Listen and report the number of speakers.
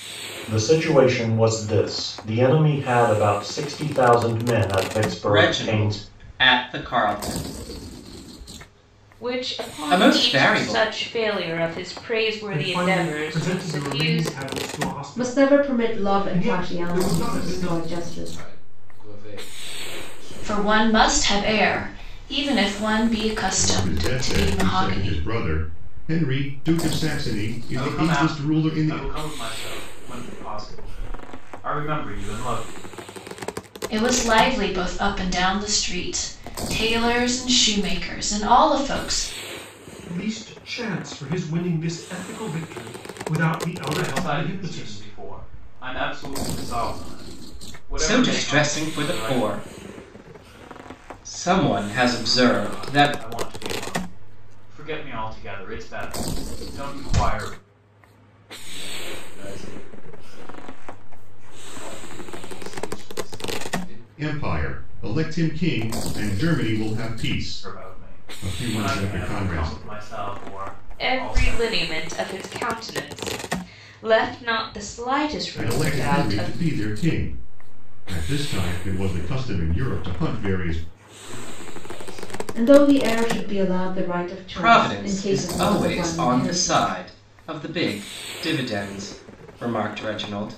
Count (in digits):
9